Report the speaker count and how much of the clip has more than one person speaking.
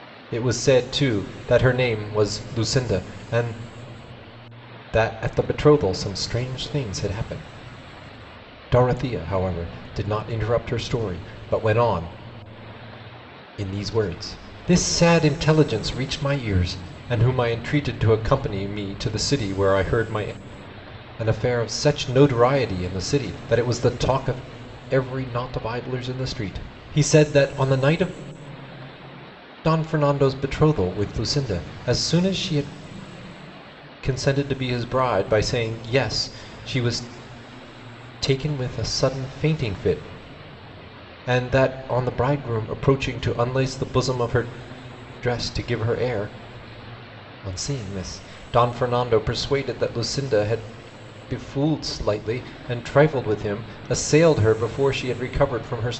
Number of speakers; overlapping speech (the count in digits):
1, no overlap